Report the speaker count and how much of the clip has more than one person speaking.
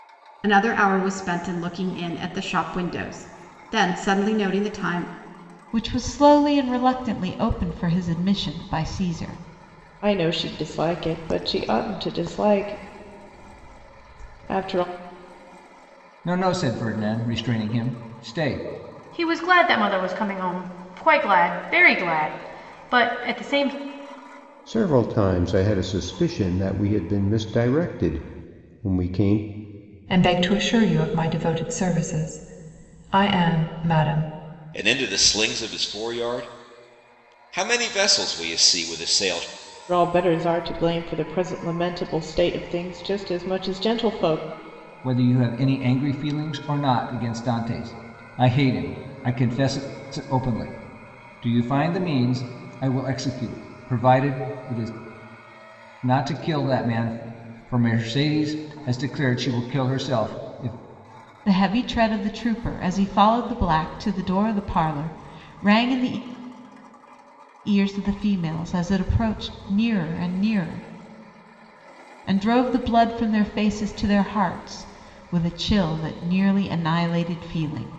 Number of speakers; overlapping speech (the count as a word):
eight, no overlap